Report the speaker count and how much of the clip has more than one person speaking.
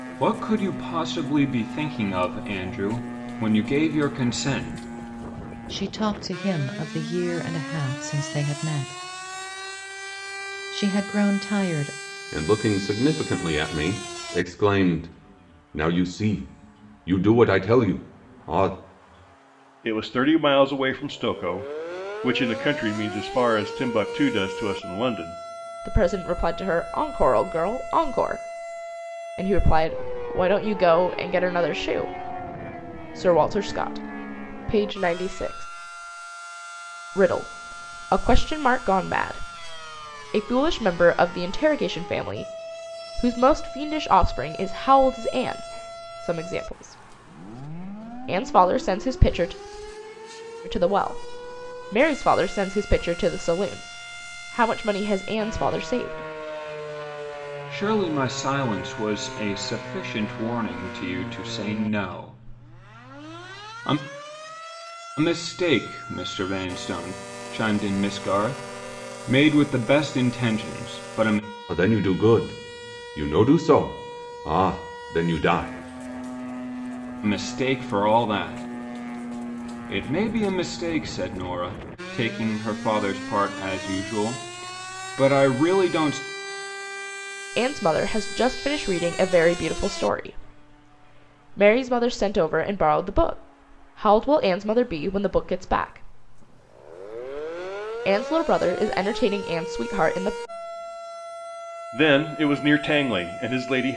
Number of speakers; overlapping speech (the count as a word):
five, no overlap